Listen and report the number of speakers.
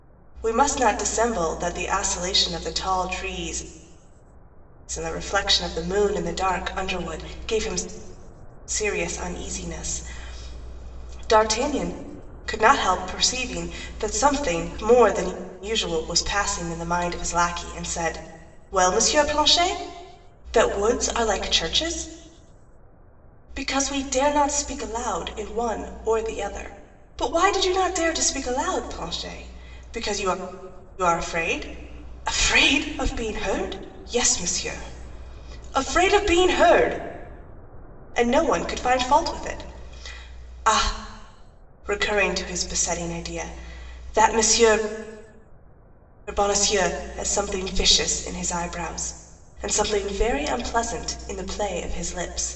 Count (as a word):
one